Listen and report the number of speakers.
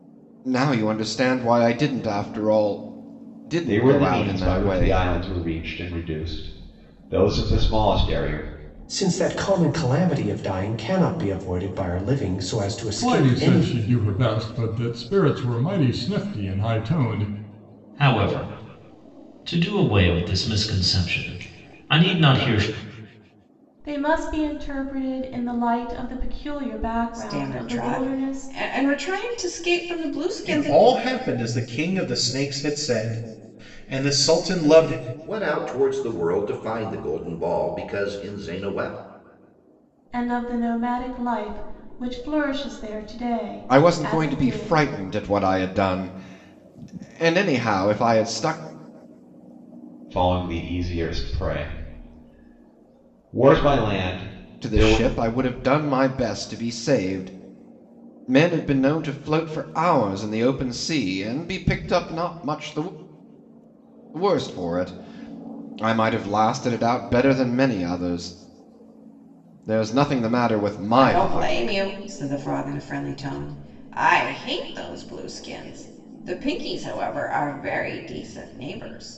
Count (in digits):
9